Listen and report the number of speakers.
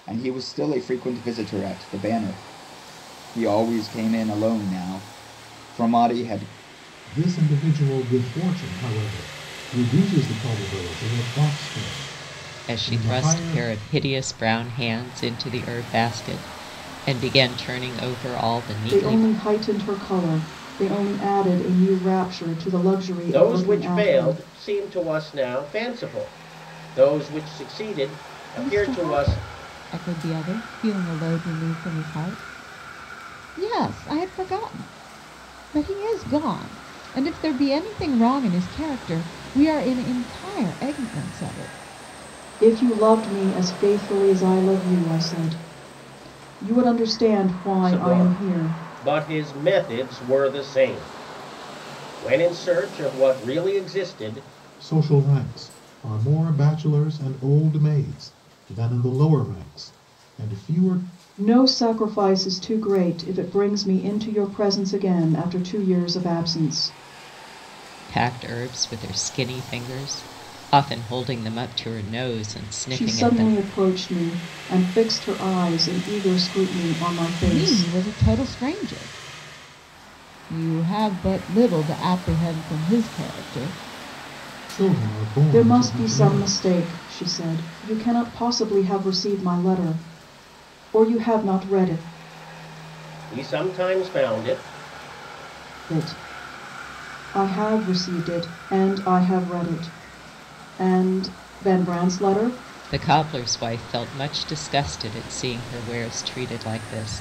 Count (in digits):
6